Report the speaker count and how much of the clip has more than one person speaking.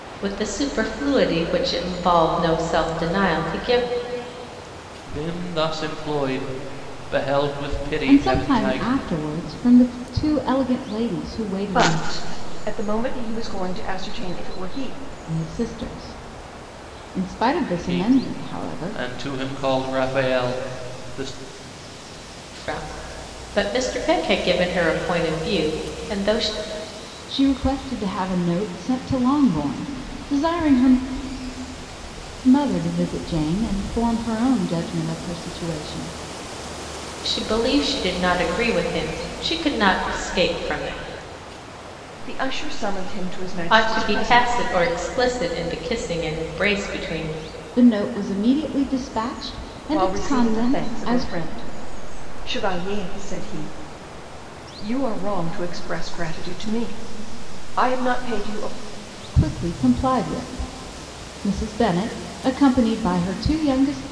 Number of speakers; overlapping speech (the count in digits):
4, about 8%